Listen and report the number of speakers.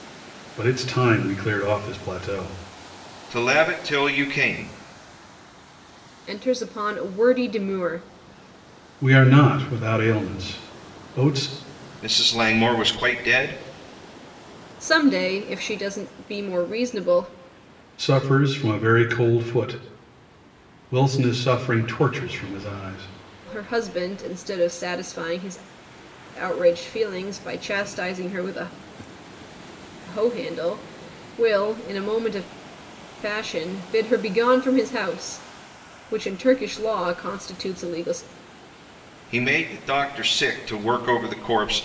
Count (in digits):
3